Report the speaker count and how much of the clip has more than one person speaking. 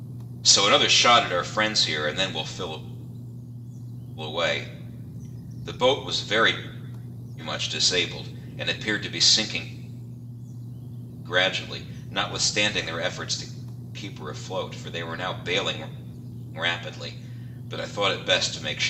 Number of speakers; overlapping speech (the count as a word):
one, no overlap